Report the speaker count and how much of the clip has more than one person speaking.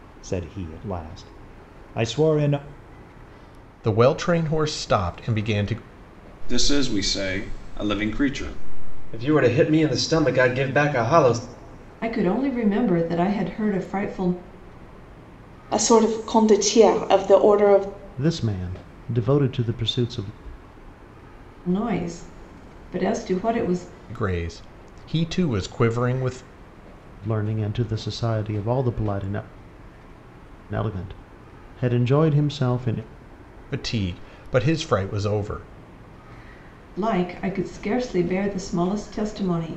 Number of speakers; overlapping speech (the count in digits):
7, no overlap